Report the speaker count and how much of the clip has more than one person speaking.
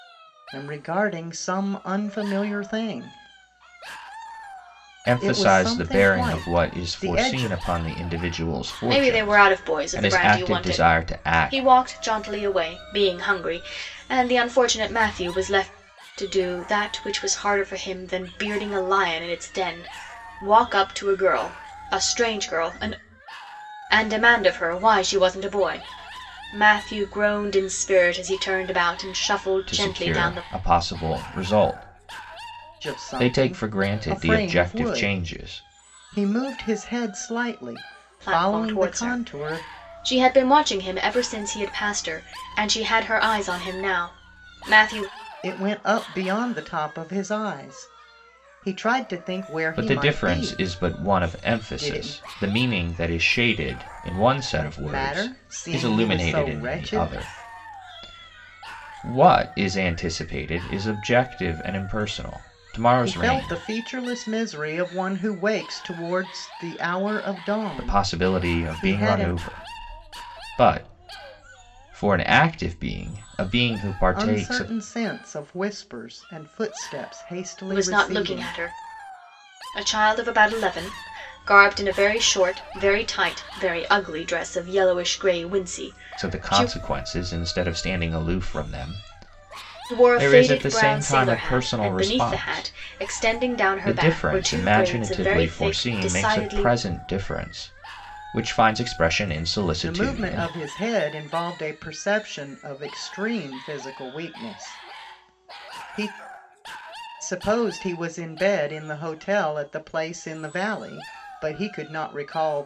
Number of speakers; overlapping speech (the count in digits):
3, about 23%